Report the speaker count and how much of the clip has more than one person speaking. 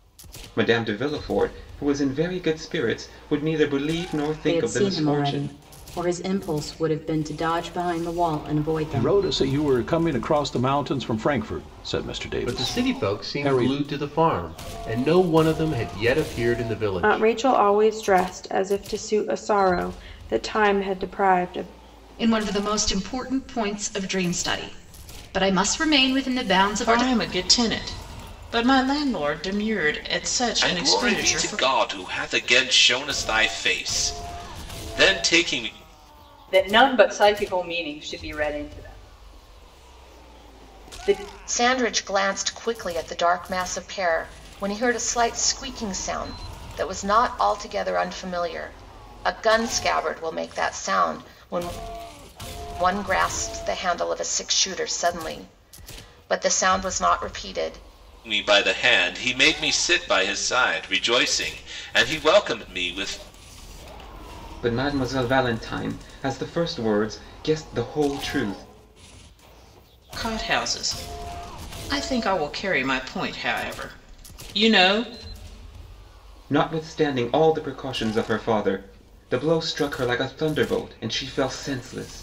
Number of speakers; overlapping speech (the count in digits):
10, about 6%